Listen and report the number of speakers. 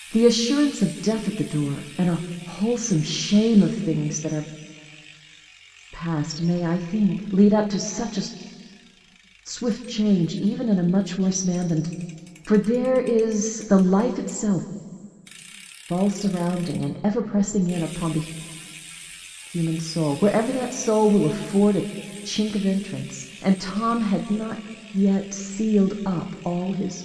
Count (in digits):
1